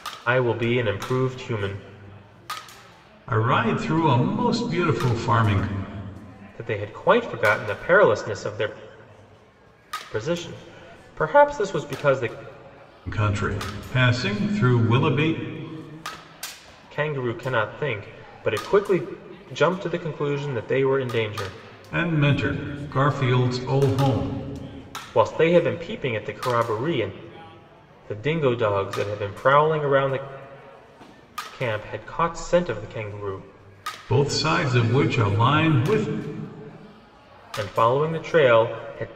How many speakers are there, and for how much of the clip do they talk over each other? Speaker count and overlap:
two, no overlap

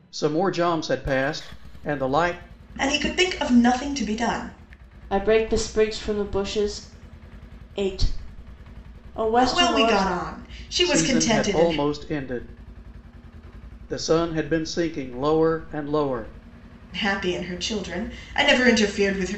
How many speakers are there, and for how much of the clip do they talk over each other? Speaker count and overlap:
three, about 9%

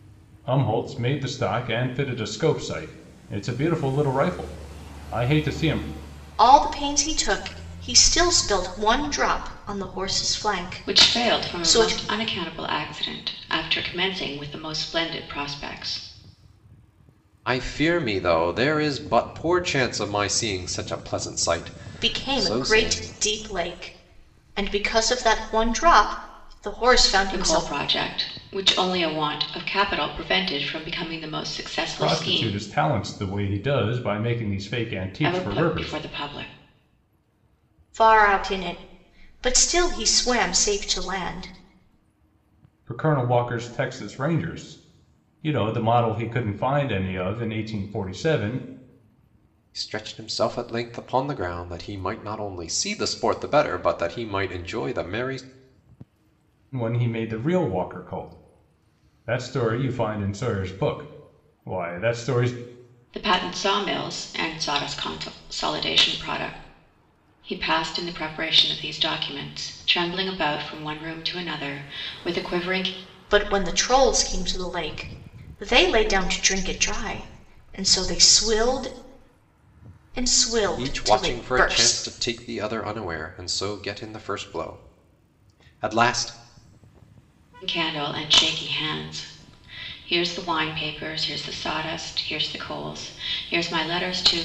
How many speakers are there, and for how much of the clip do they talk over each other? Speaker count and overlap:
four, about 6%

